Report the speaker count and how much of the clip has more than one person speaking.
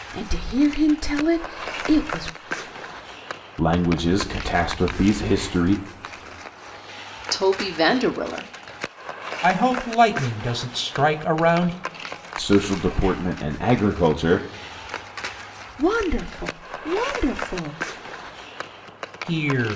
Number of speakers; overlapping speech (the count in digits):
4, no overlap